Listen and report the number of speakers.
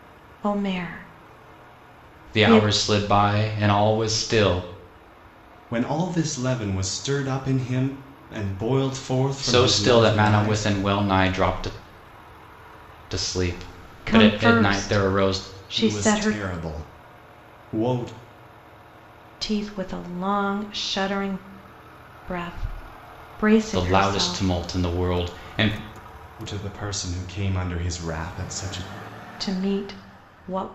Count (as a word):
three